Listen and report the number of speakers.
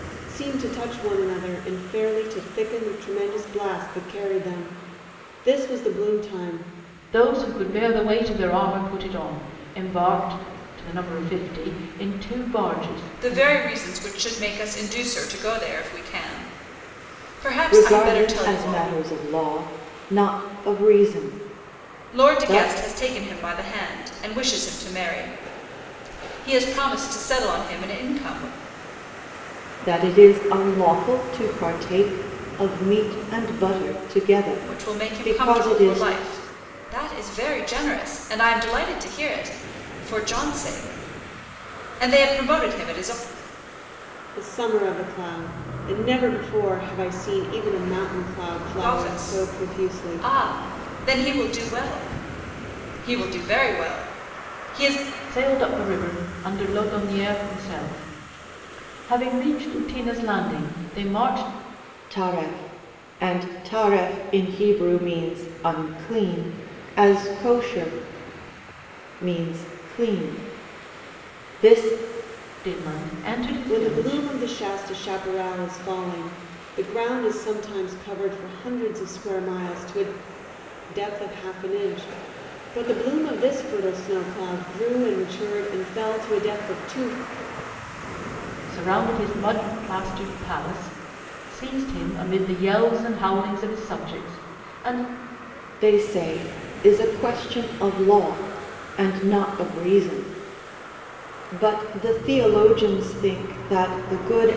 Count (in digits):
4